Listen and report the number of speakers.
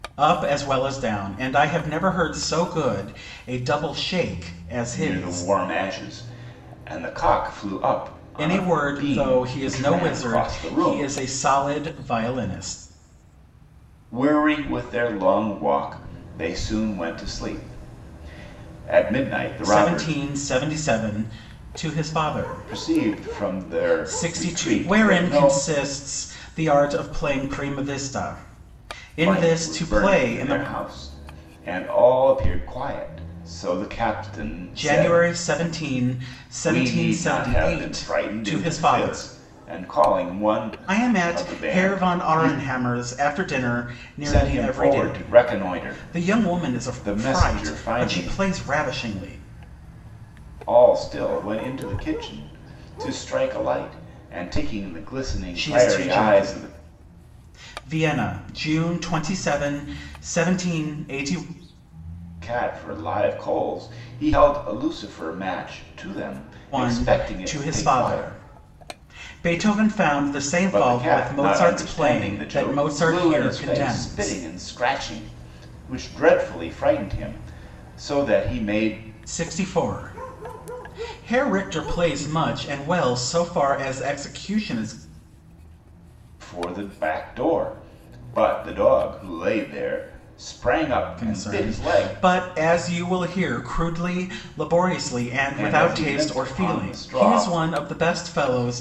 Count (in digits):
2